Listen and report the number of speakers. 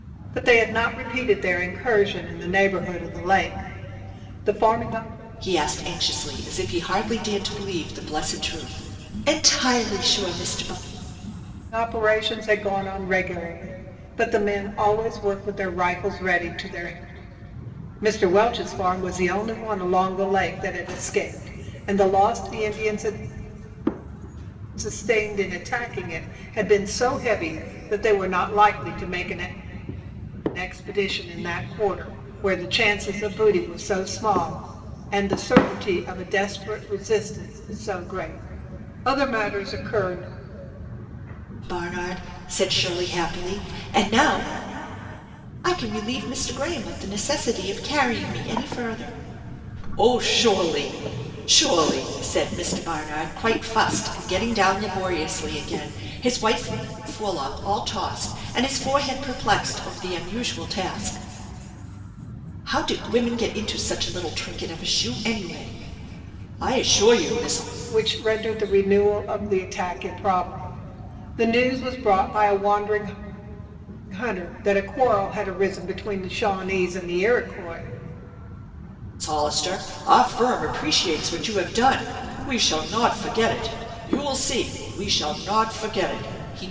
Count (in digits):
2